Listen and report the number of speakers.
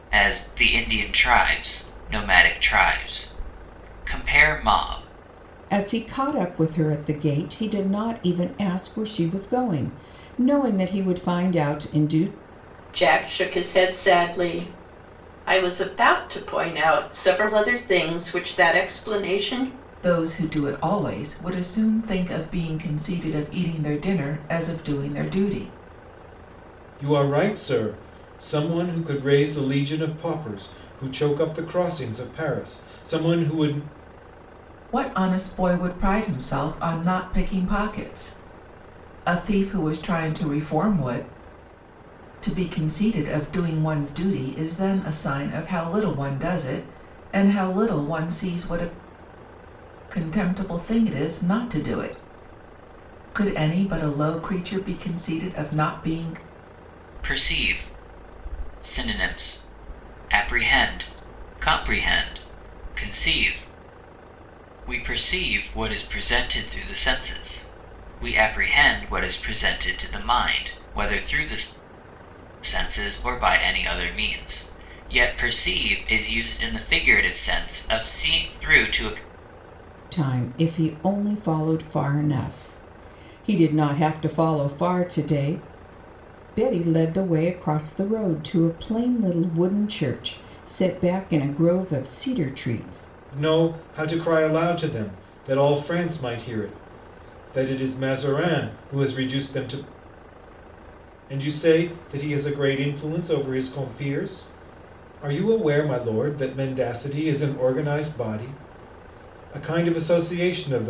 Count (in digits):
5